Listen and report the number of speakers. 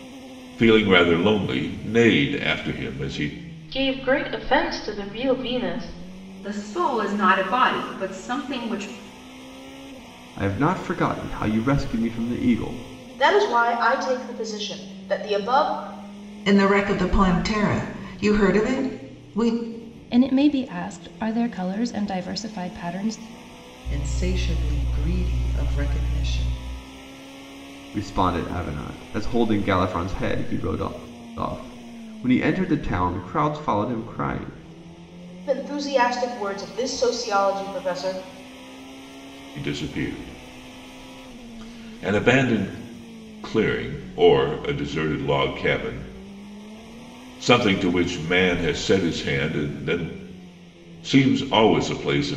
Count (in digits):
8